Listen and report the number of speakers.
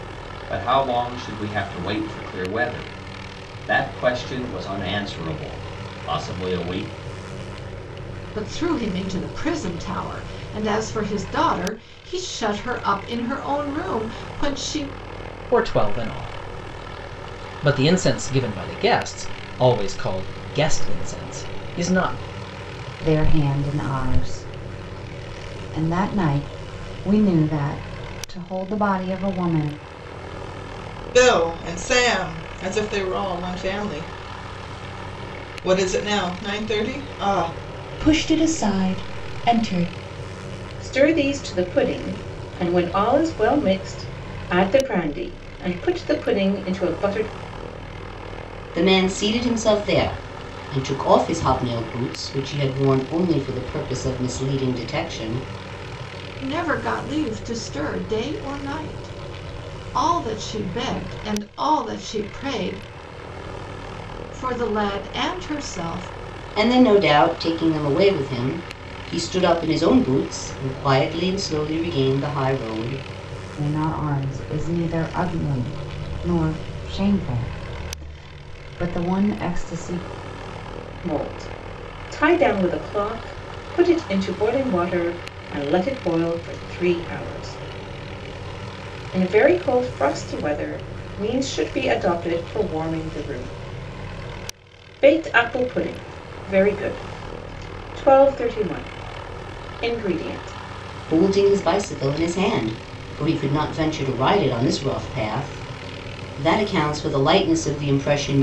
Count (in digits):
8